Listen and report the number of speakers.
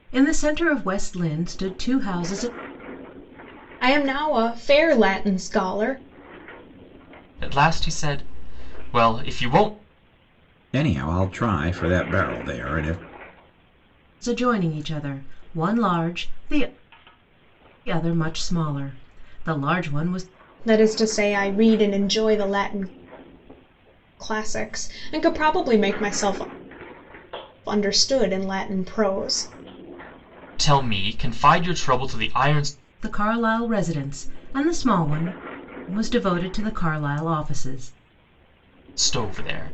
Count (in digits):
4